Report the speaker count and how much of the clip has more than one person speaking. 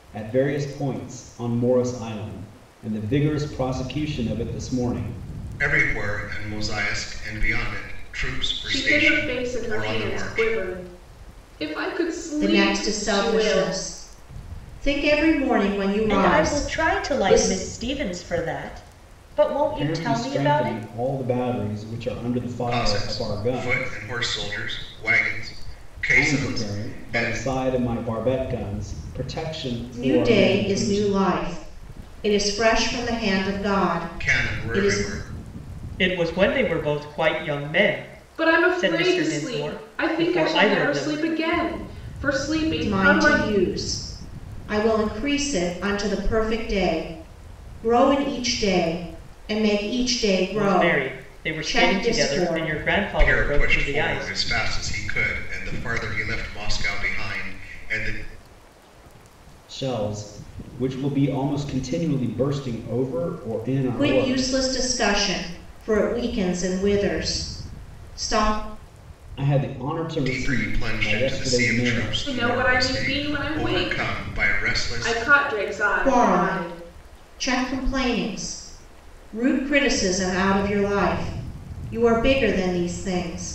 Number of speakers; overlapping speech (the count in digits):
5, about 29%